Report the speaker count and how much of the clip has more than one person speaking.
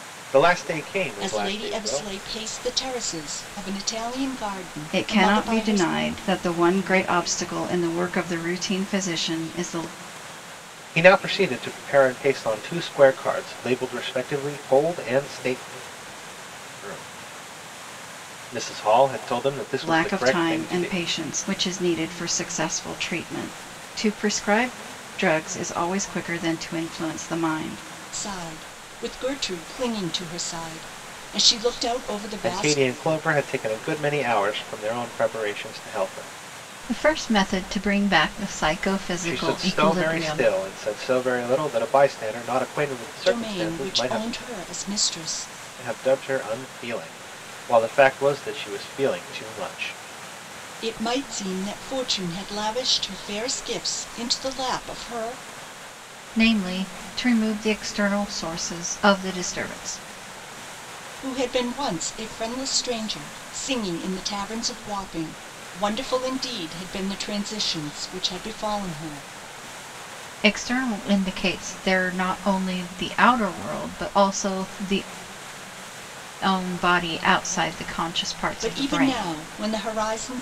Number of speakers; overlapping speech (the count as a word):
three, about 8%